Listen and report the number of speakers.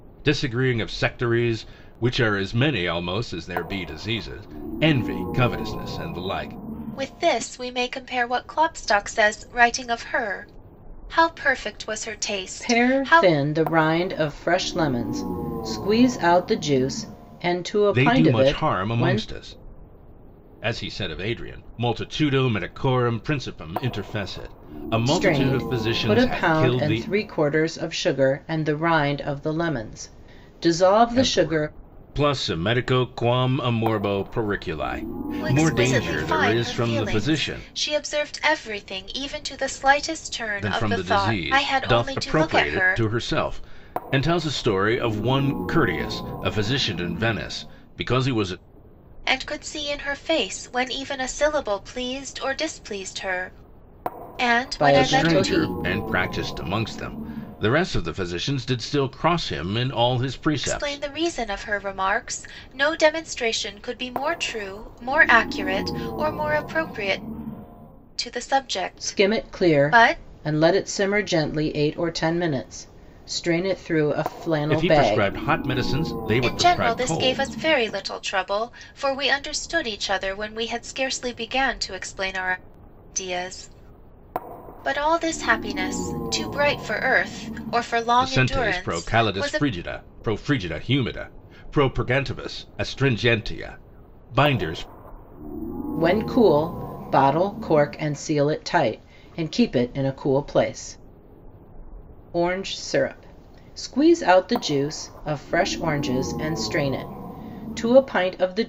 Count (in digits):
3